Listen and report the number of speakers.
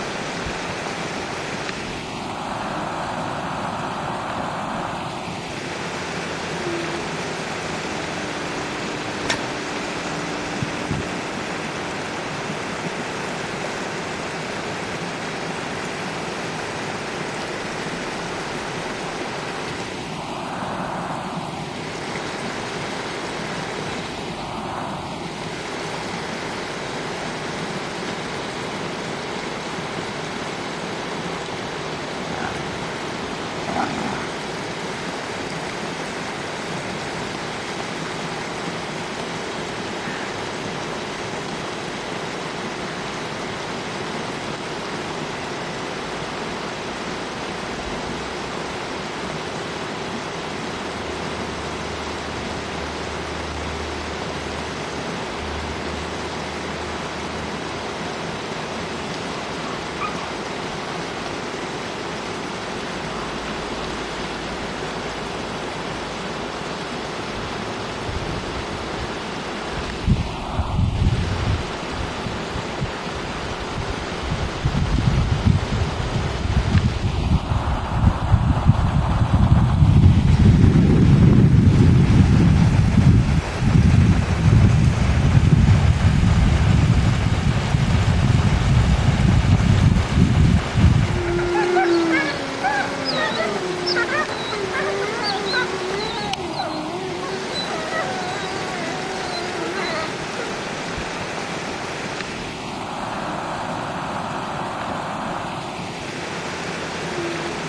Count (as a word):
zero